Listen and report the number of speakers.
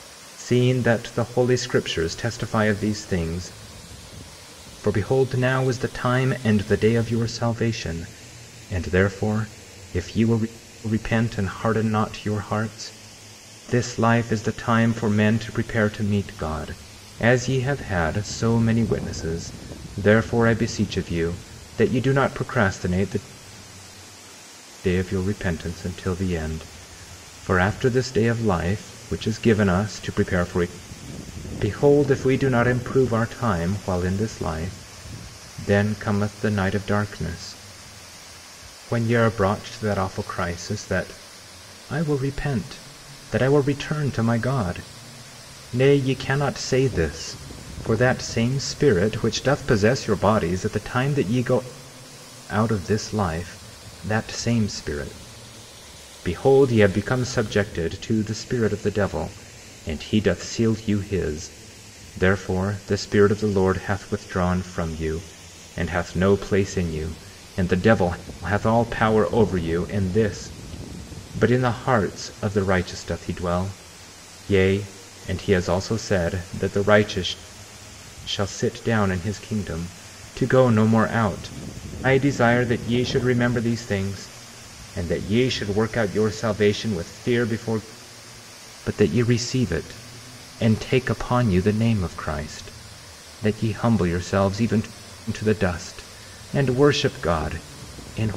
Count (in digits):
1